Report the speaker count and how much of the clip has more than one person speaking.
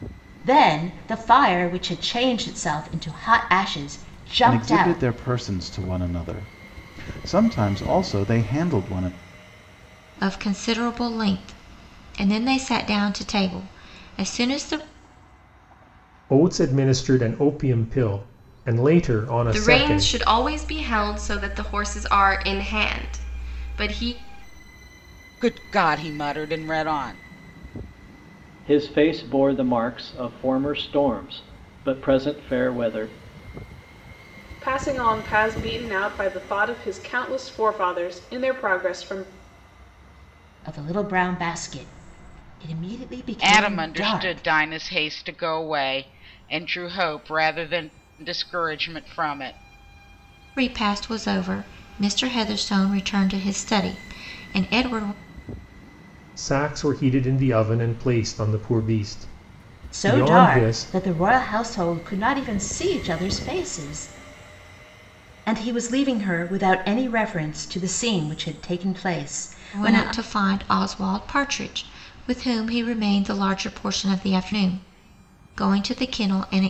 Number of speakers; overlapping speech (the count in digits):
8, about 5%